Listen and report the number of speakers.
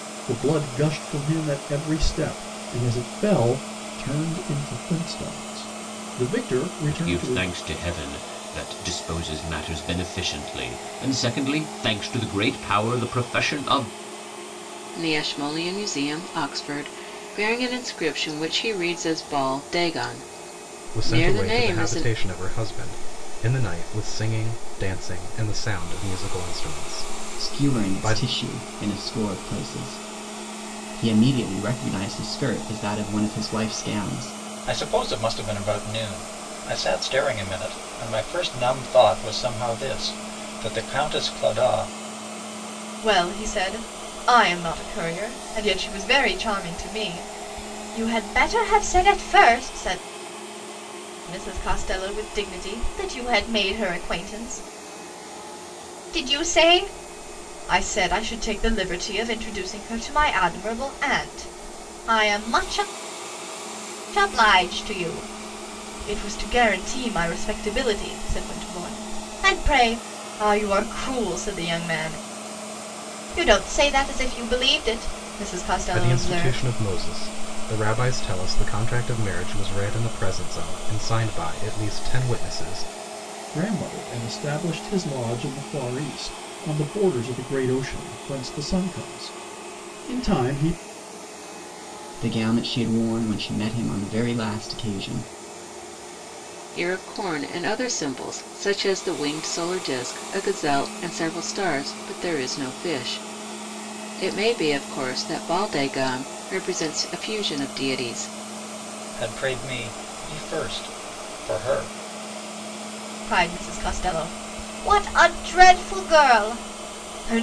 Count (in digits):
7